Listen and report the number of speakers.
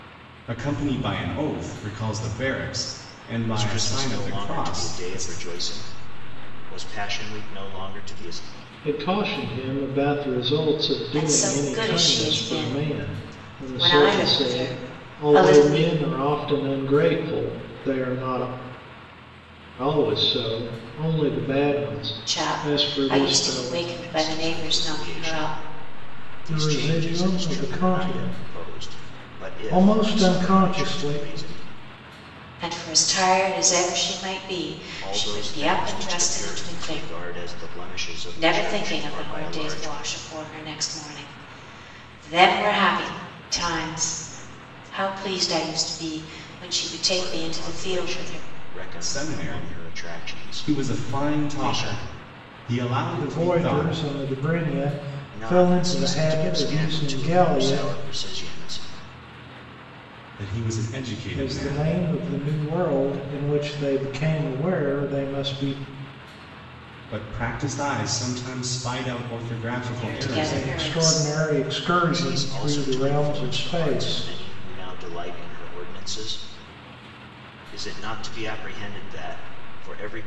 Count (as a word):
four